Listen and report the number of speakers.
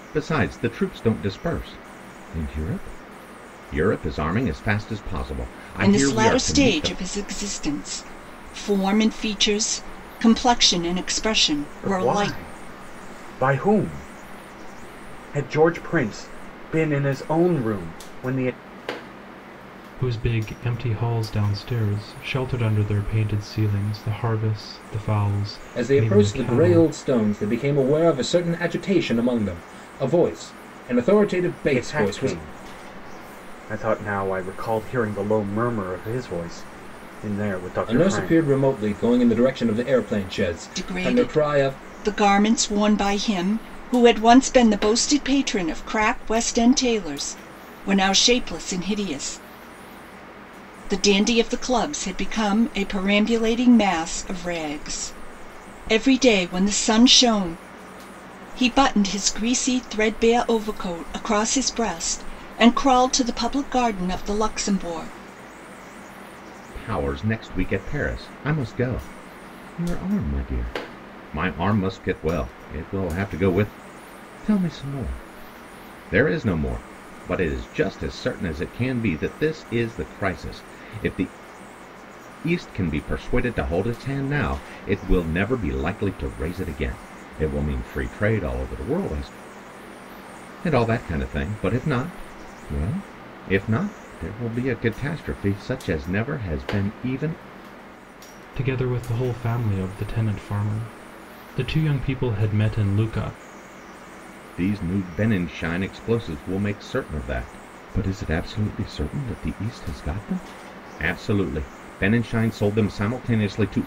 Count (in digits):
5